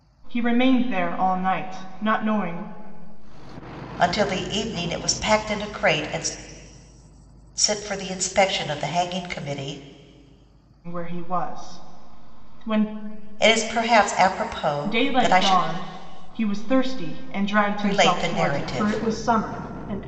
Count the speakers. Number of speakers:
2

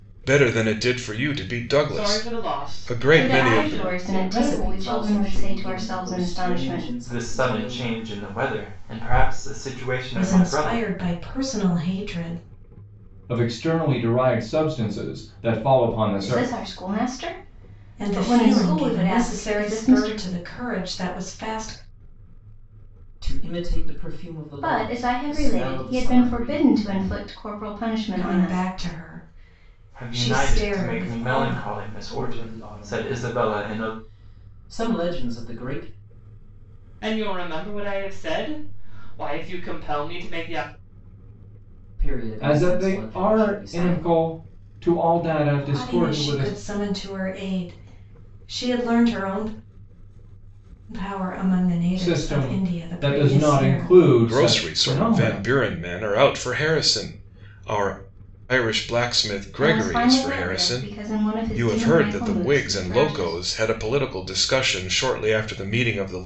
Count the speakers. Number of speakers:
7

